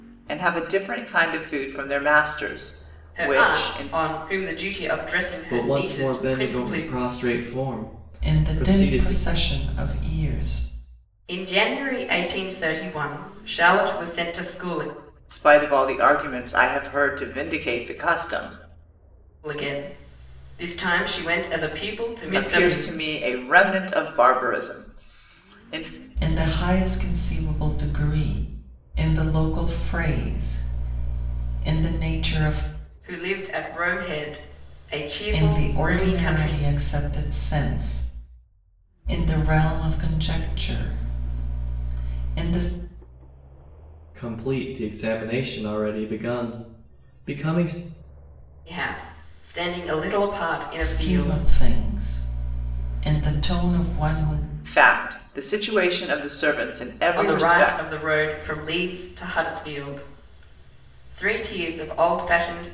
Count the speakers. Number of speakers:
4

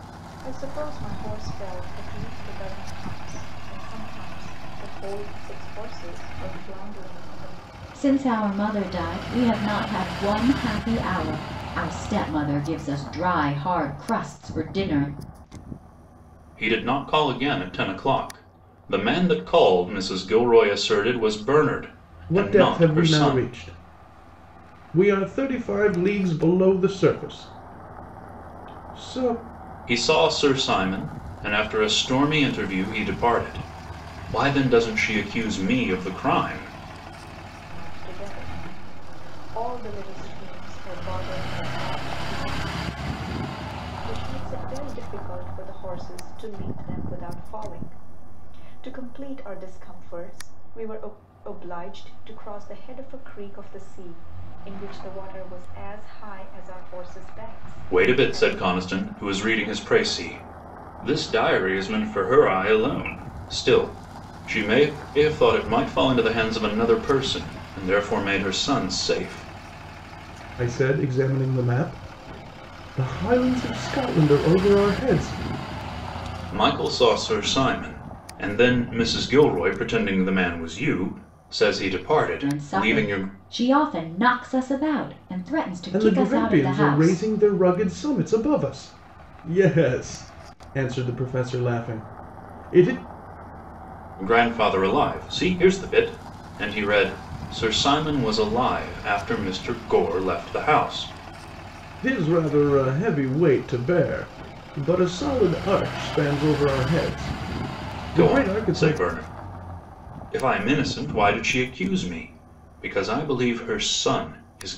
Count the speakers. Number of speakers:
4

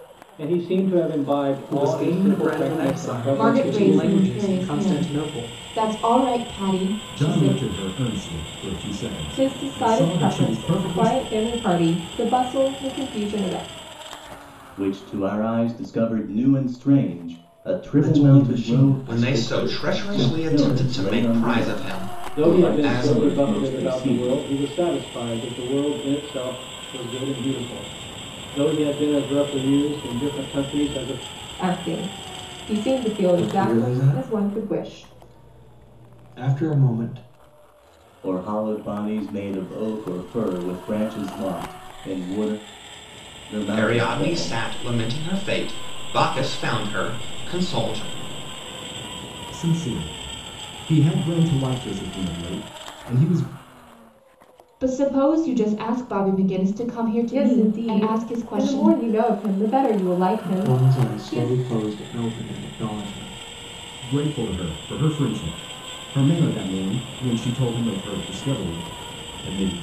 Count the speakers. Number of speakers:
8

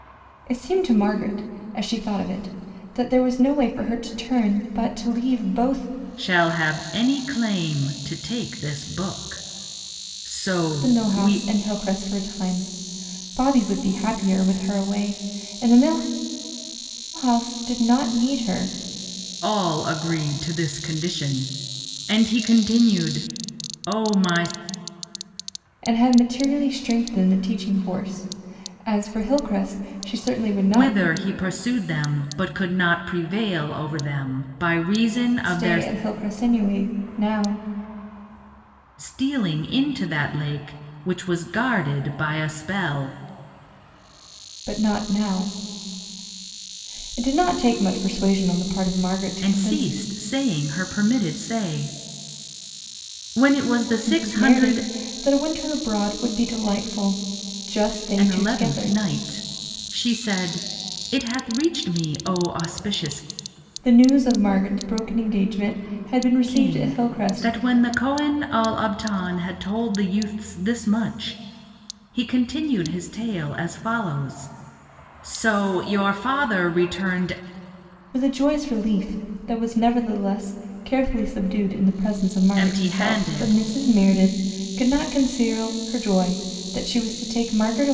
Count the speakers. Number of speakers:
2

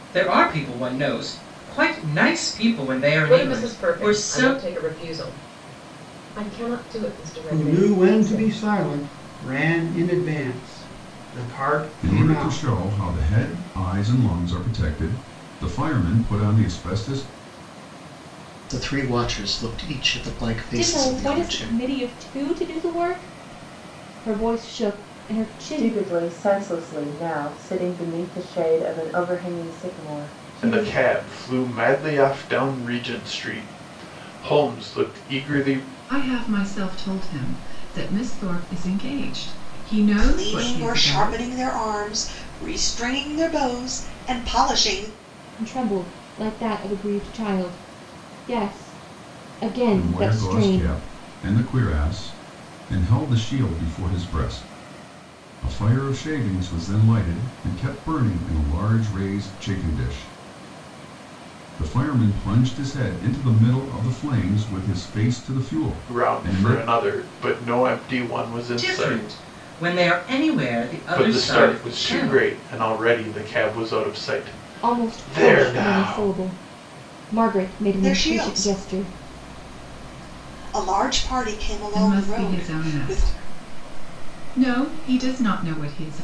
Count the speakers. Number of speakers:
10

